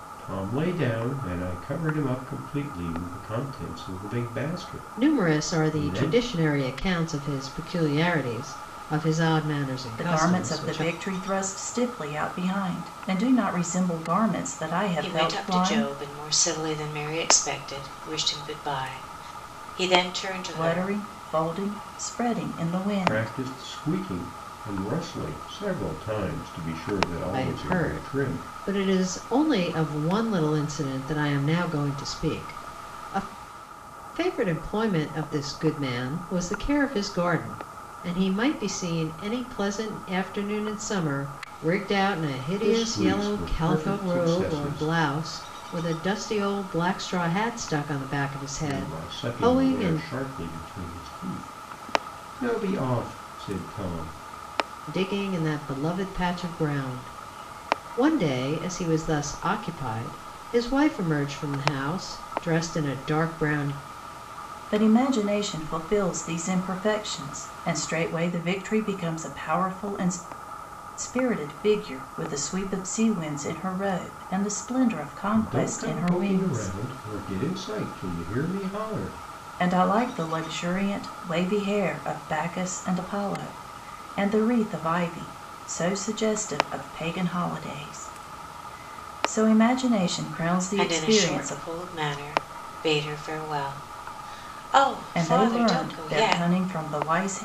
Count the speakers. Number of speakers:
4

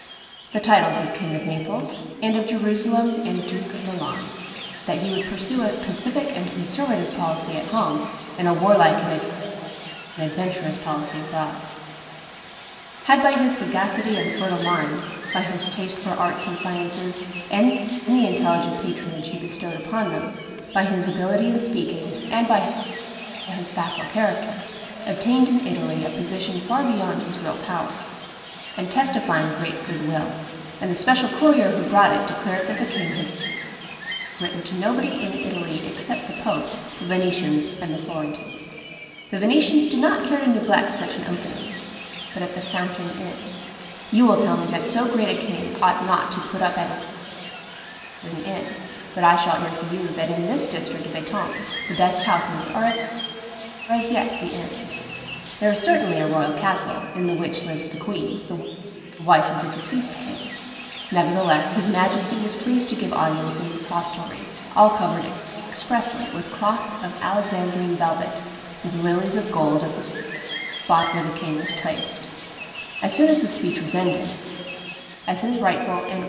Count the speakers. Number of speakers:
1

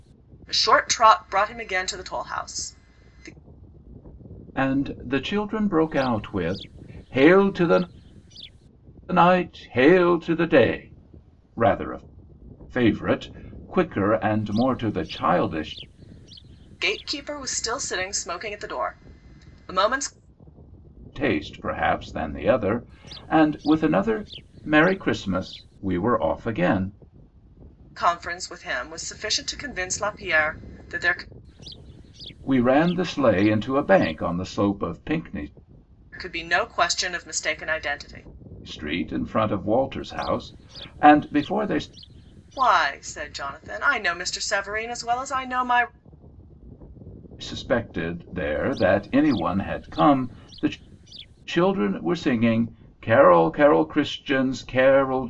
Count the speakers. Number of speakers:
2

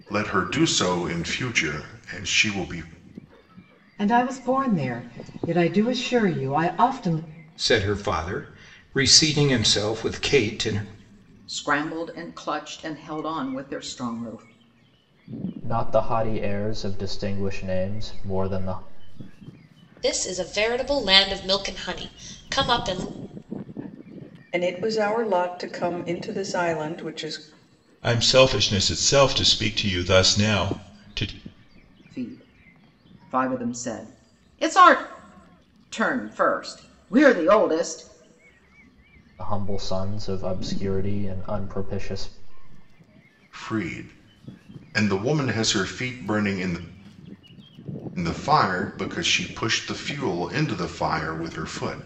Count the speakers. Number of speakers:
8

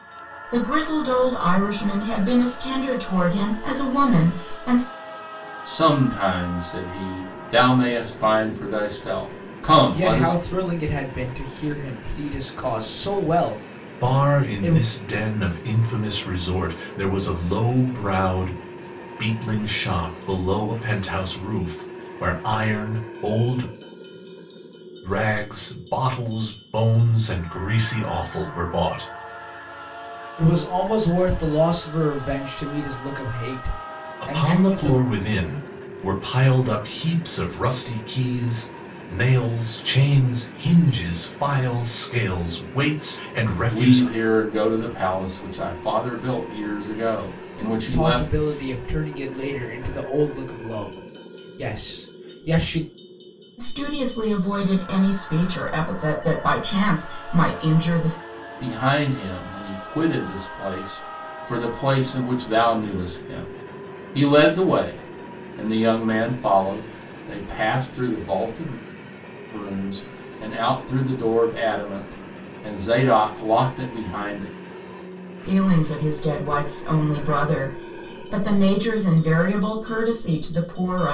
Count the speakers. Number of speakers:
4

